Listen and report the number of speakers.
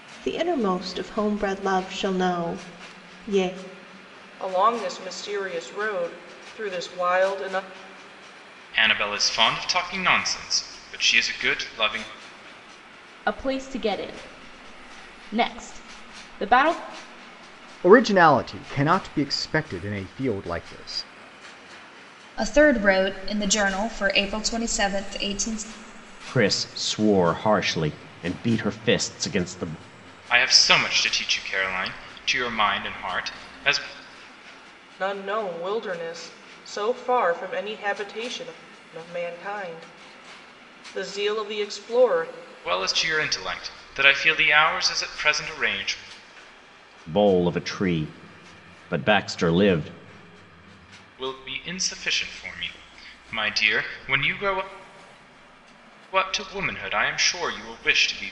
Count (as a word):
seven